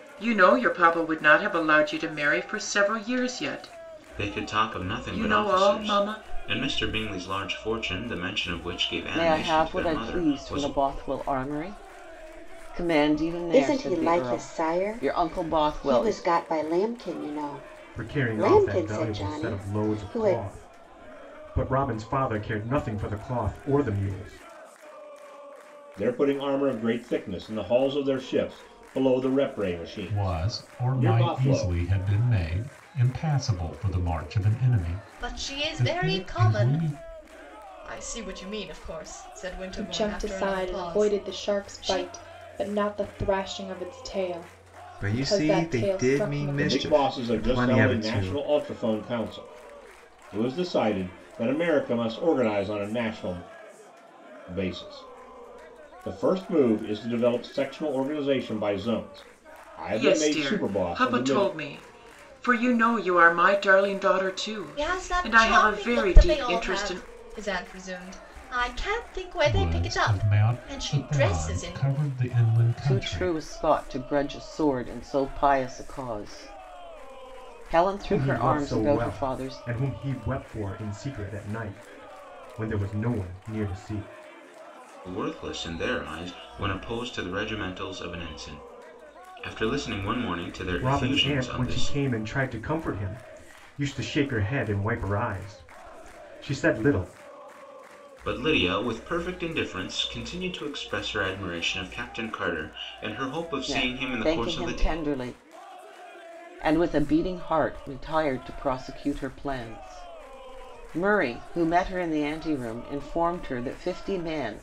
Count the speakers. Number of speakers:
ten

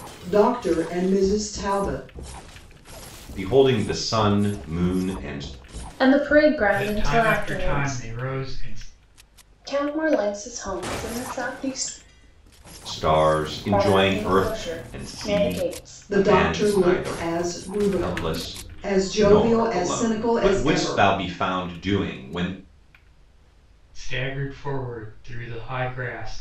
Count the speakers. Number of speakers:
four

